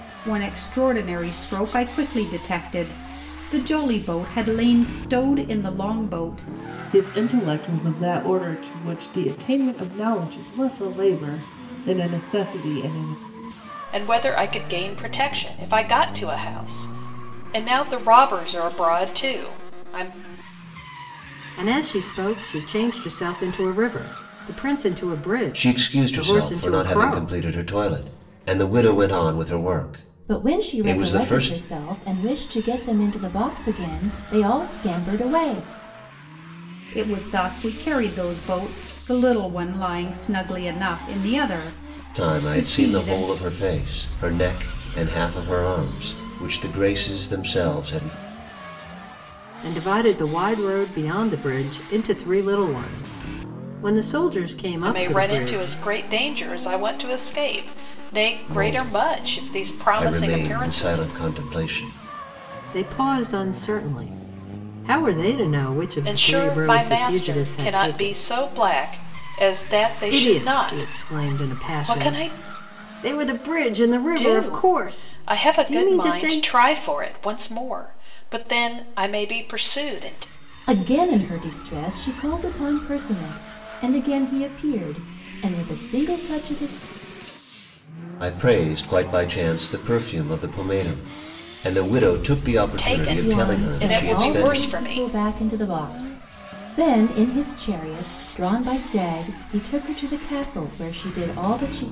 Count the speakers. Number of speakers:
six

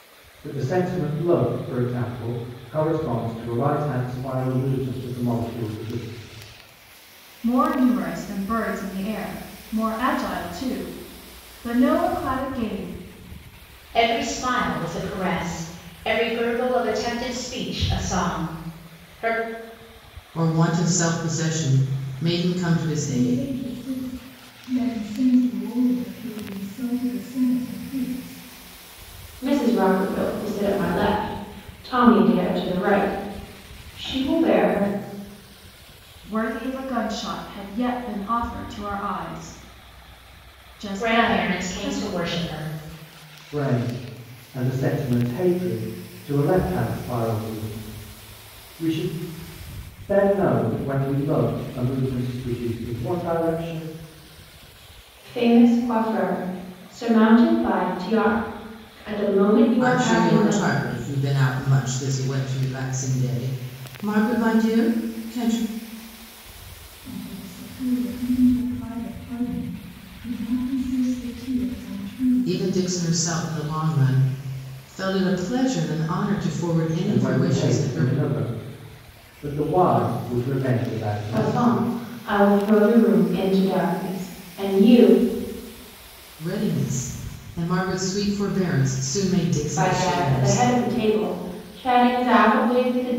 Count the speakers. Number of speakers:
six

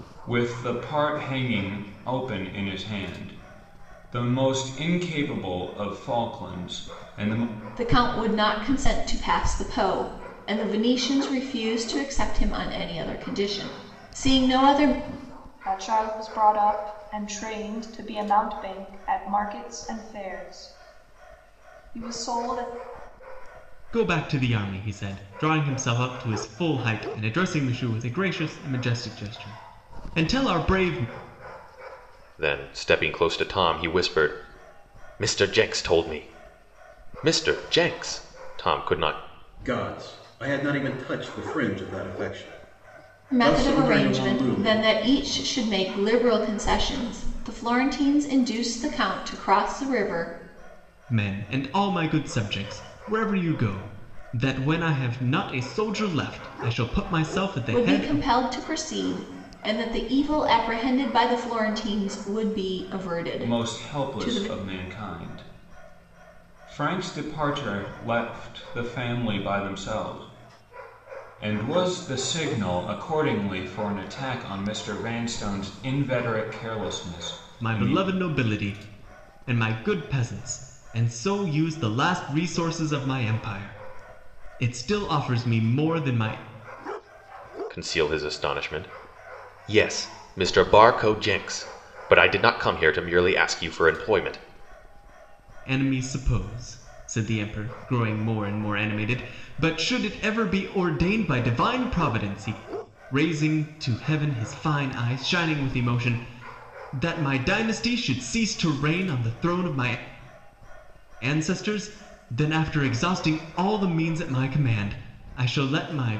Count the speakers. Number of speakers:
six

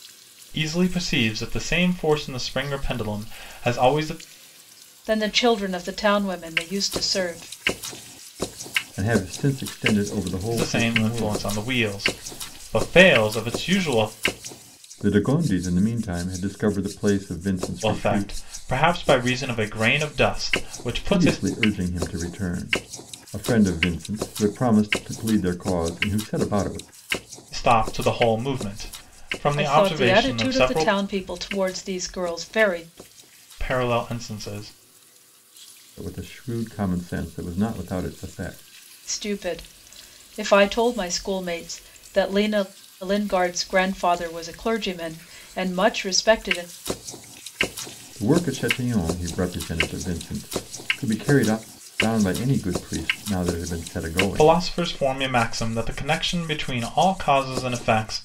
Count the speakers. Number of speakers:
three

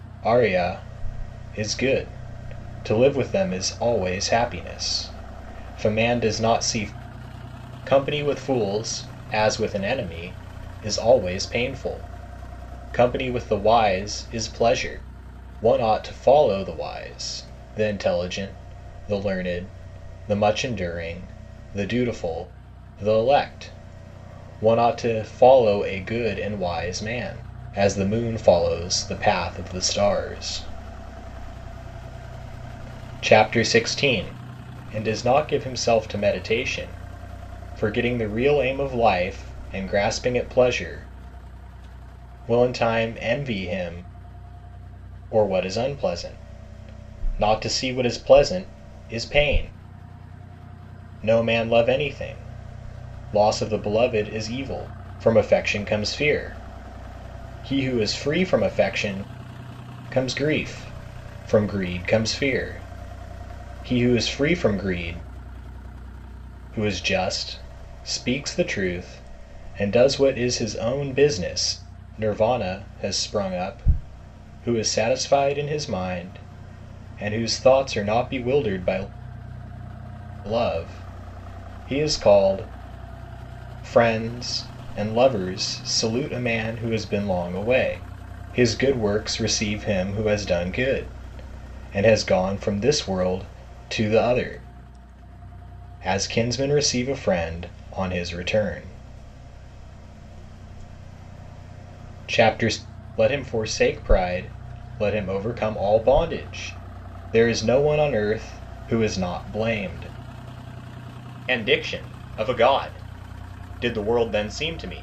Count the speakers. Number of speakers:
one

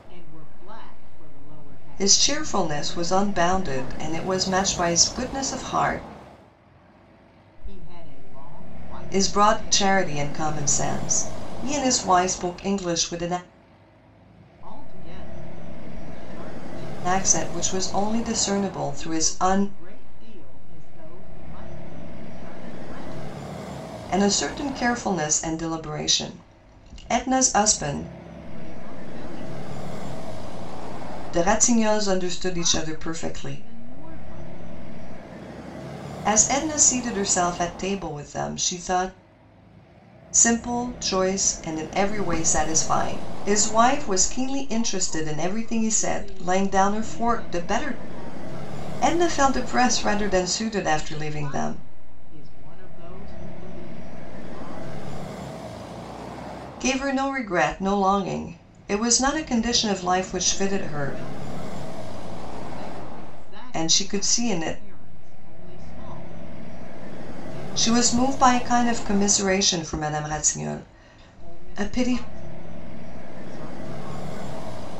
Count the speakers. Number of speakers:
two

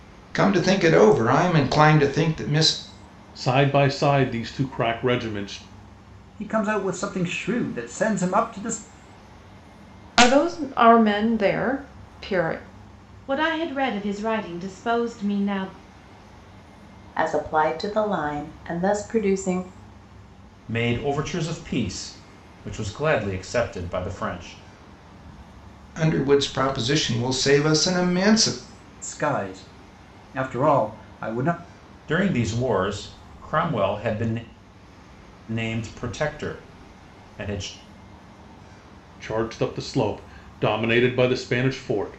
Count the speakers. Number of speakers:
seven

